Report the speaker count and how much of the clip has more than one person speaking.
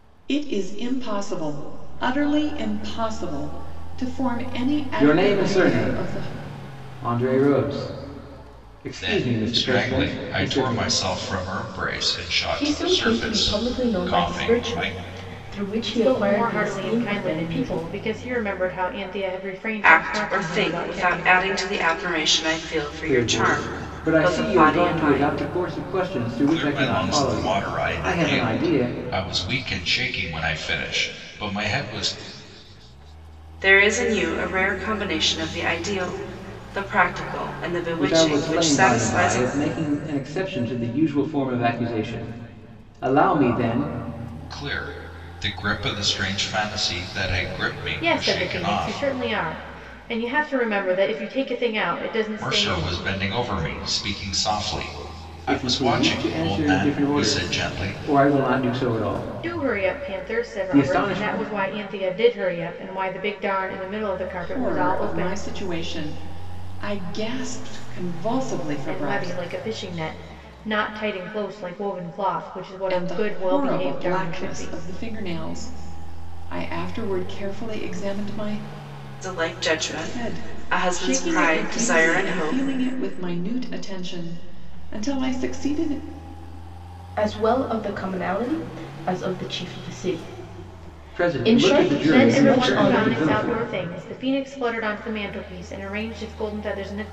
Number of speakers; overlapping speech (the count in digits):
6, about 32%